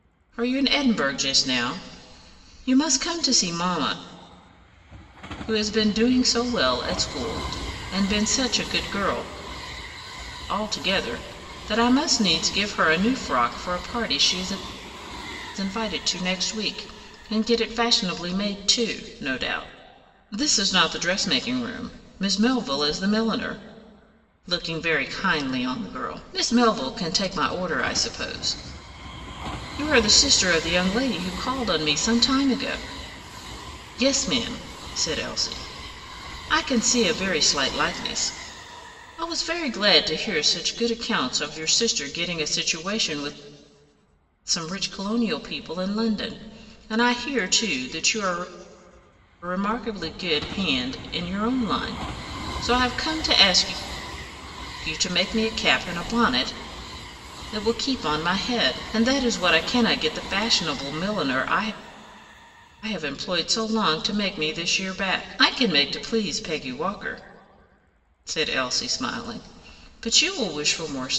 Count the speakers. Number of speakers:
one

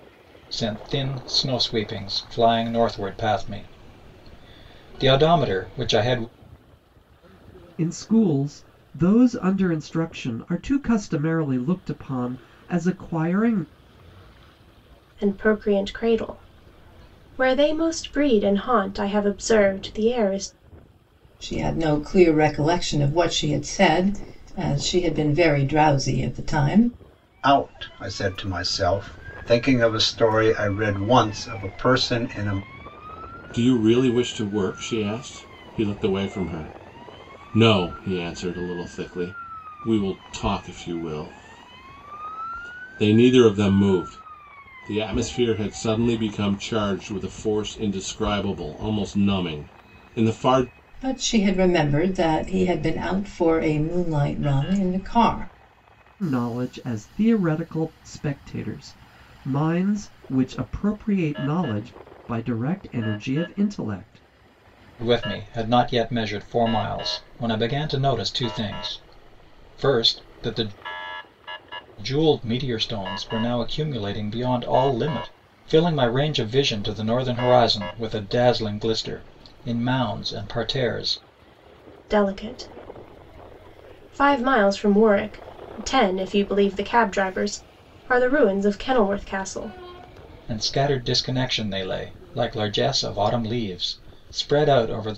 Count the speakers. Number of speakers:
six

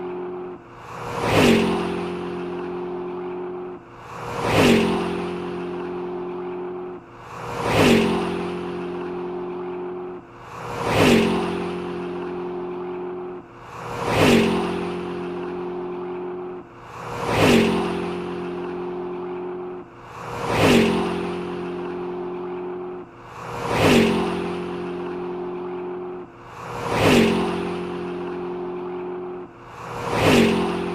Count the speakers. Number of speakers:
zero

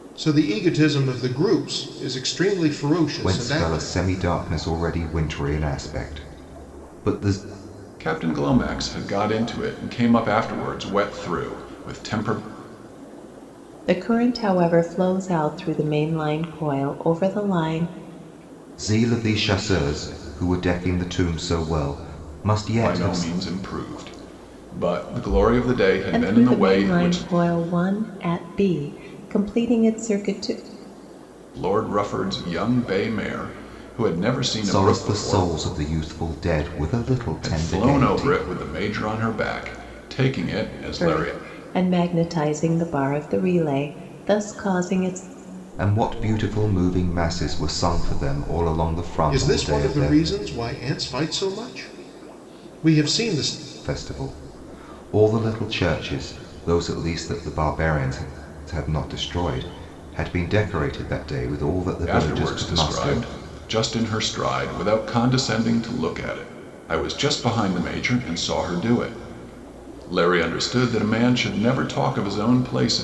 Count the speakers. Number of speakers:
four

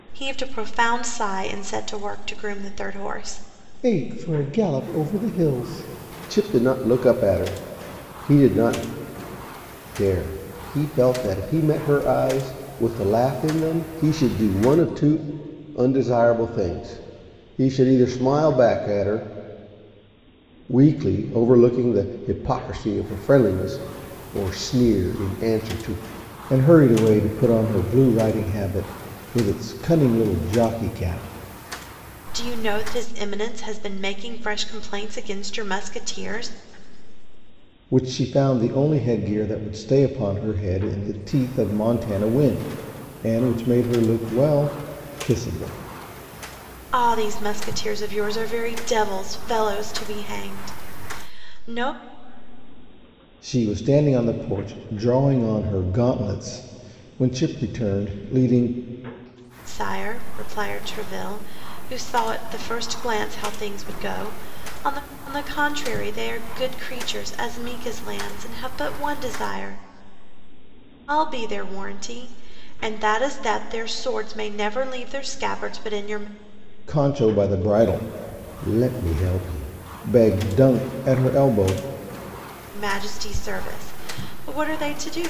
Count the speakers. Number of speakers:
two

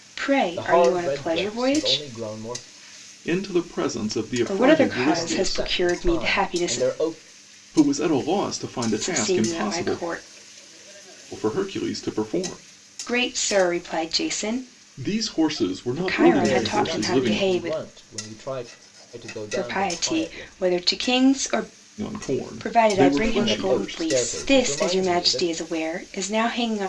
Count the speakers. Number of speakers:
three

